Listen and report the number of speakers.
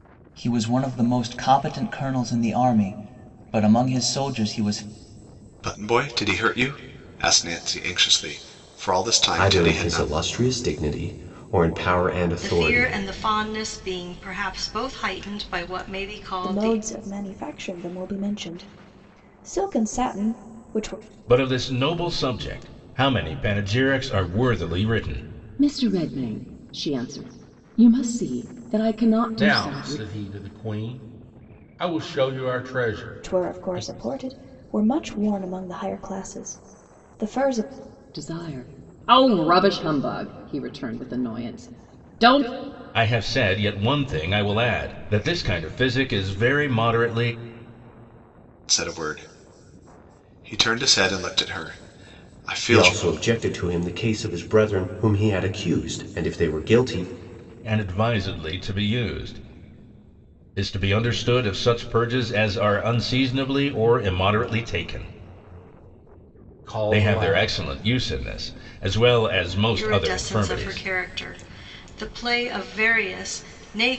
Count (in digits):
8